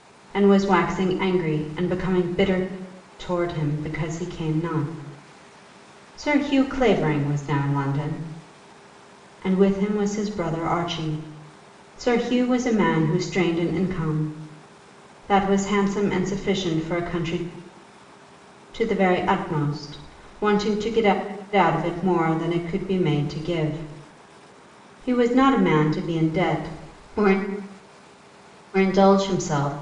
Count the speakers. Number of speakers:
1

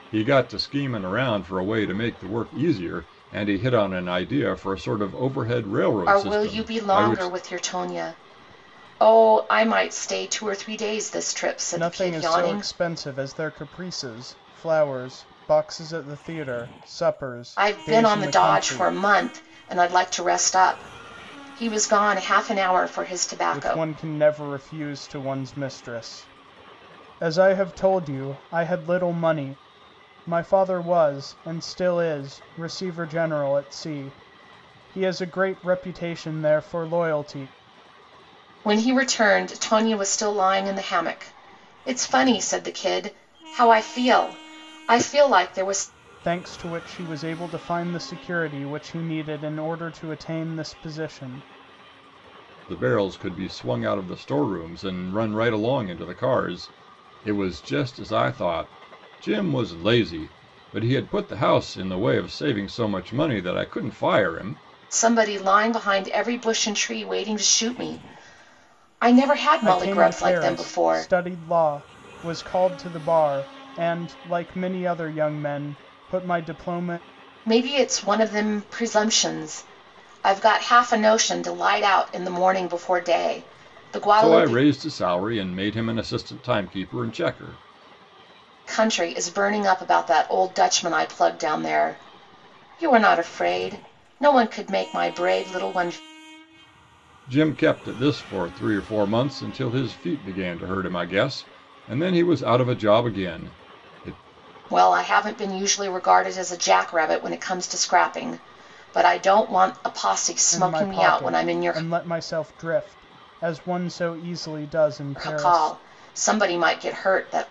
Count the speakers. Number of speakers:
3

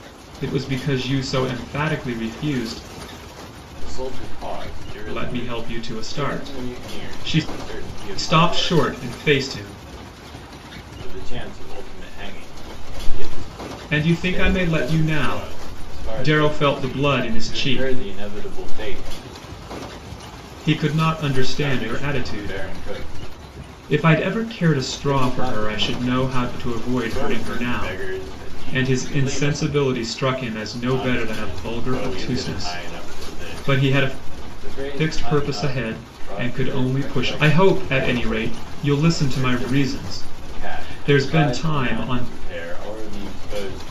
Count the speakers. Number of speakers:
2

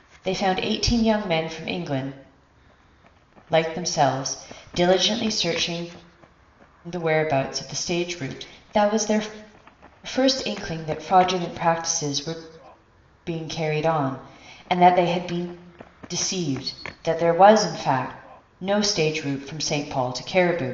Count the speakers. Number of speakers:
1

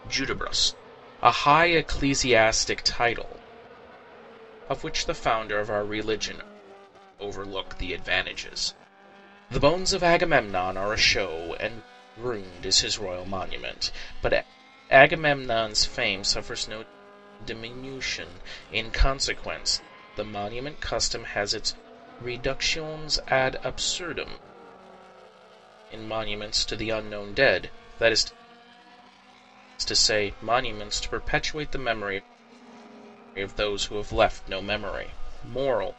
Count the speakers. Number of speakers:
1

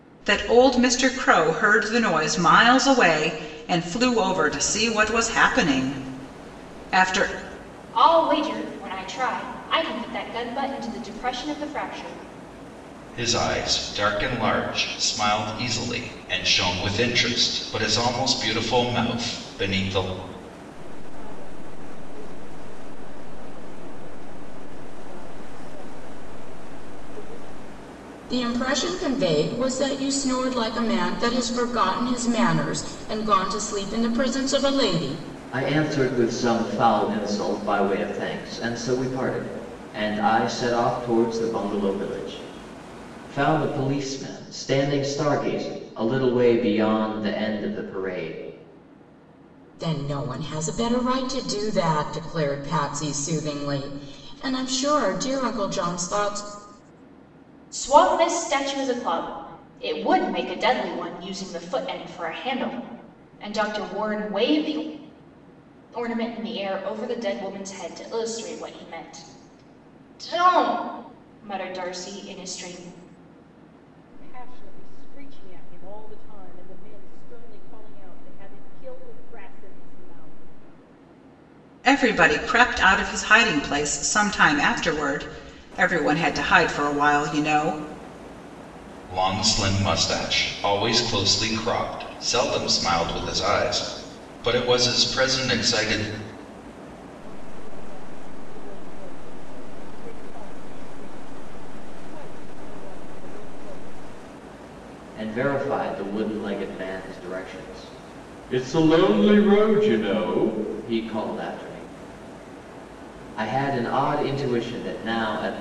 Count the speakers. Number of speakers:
6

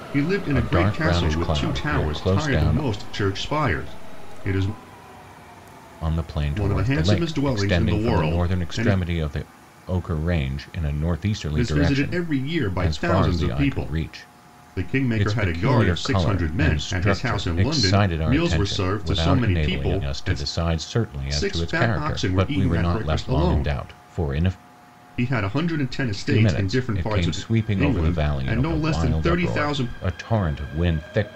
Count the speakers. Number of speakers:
2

